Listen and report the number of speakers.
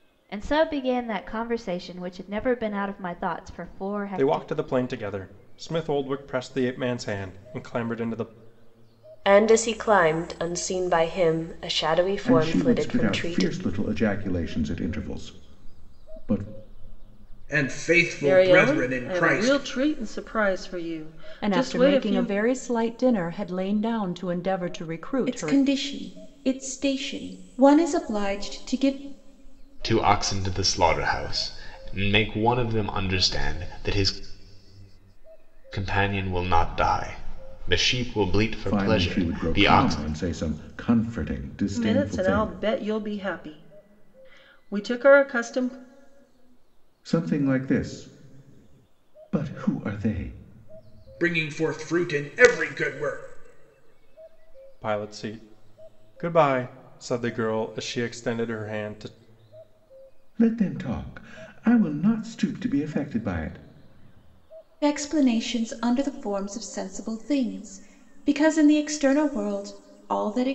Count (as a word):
nine